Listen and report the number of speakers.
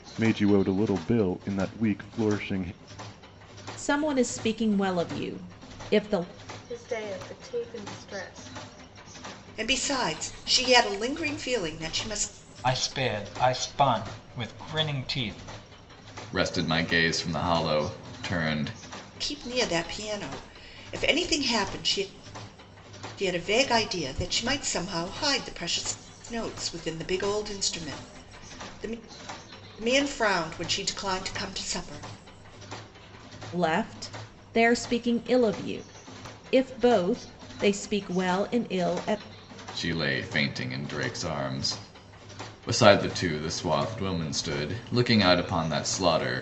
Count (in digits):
6